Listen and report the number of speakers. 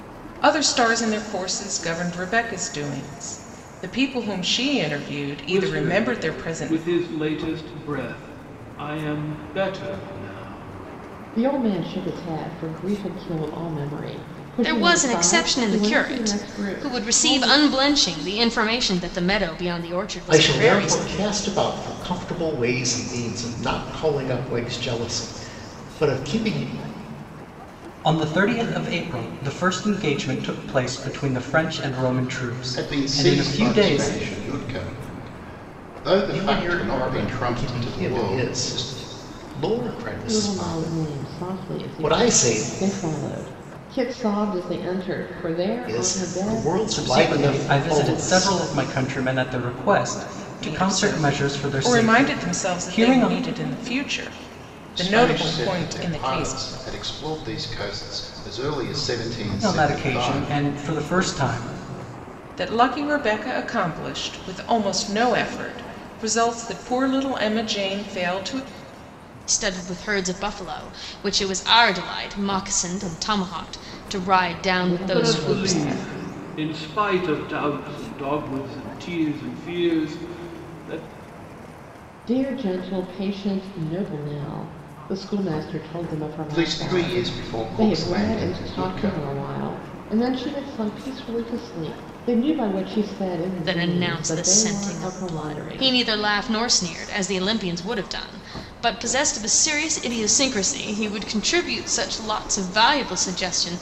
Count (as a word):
seven